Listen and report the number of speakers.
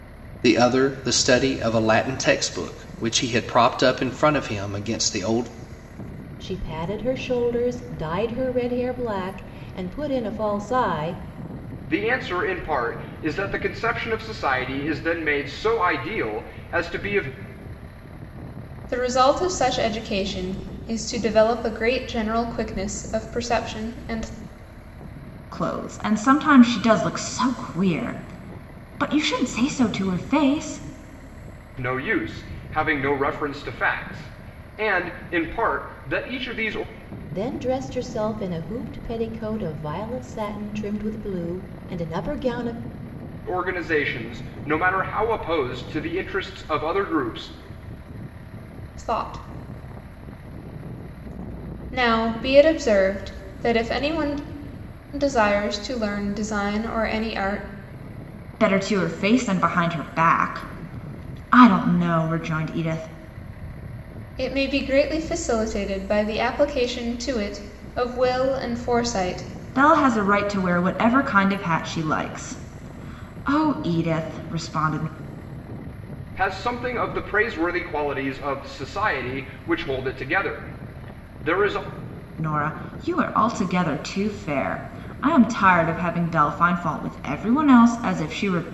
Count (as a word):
five